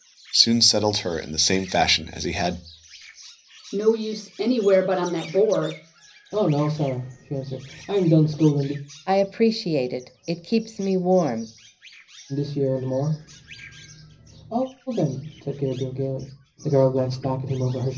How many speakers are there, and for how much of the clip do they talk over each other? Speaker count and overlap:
four, no overlap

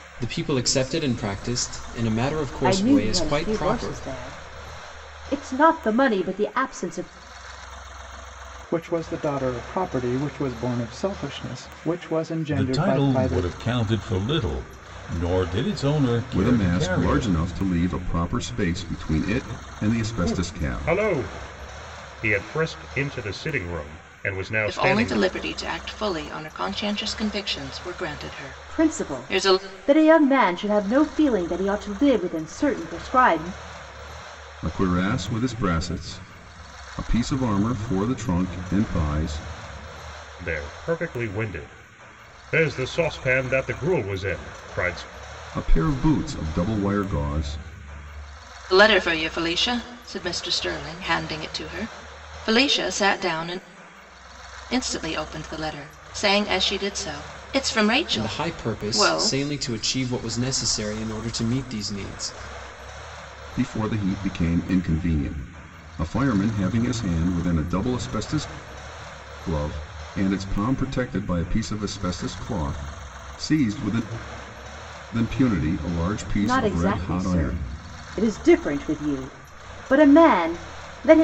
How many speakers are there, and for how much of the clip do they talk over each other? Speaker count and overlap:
seven, about 10%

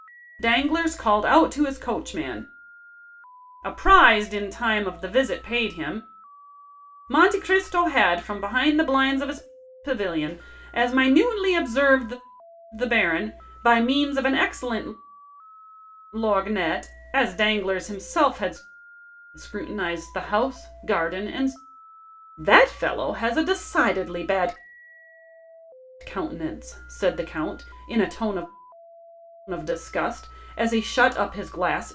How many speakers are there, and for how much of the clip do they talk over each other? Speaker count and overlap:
one, no overlap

